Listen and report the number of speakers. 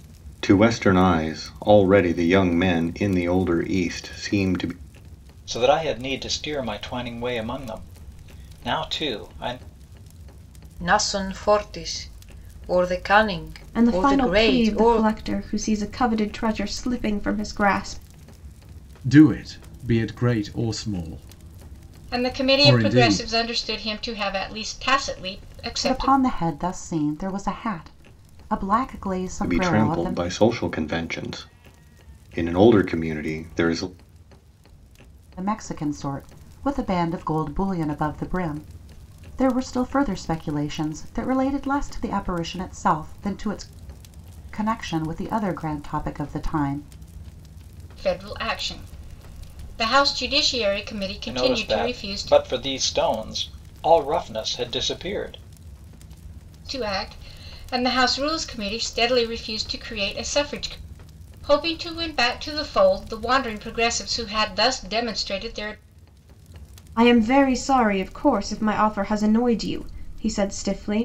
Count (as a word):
seven